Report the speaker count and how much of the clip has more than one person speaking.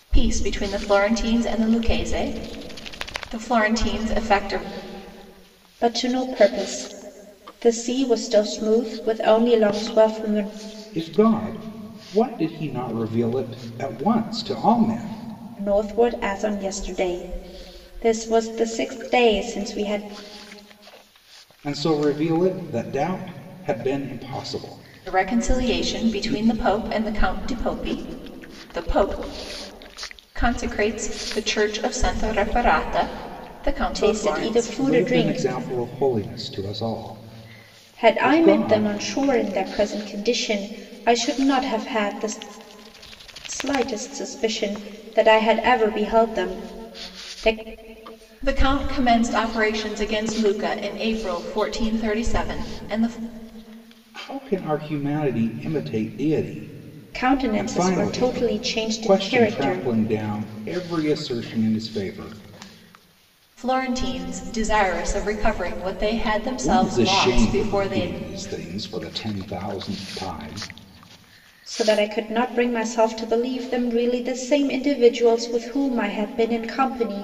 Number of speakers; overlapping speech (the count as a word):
three, about 10%